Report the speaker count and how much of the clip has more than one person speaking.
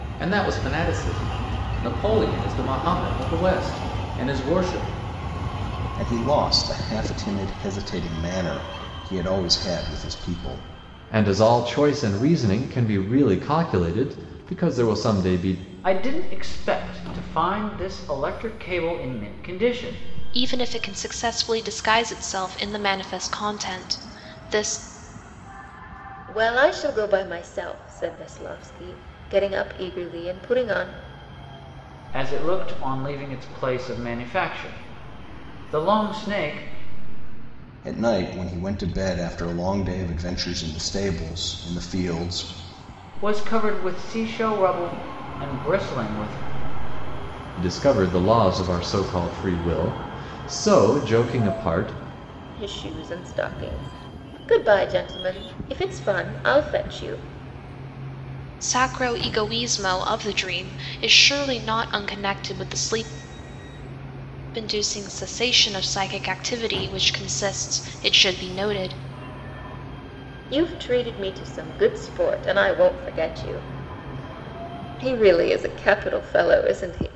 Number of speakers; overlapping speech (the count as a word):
six, no overlap